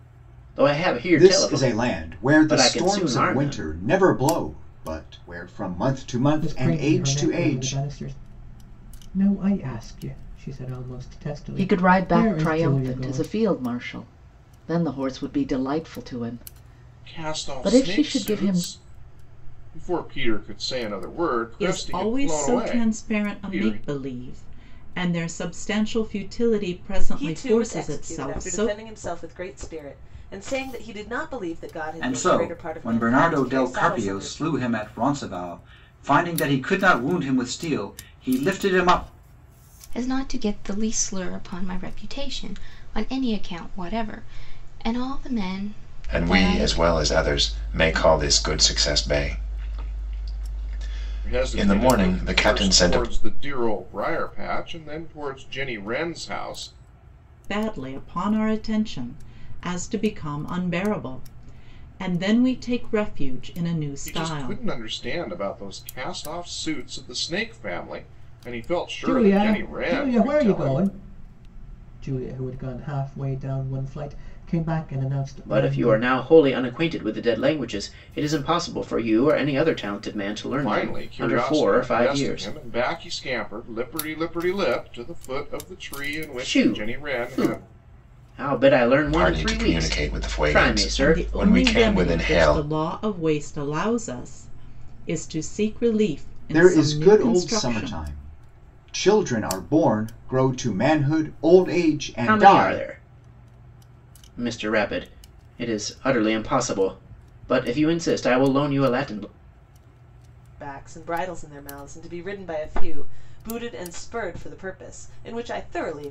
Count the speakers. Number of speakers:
ten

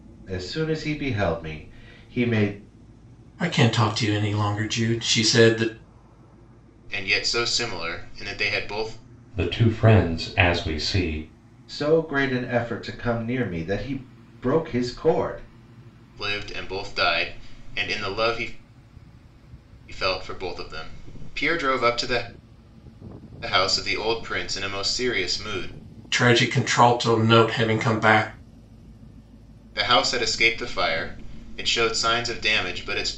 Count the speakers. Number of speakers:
four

